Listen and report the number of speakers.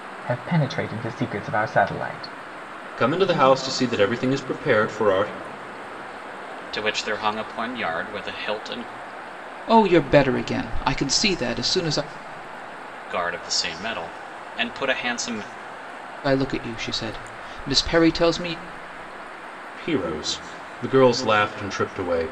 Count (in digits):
4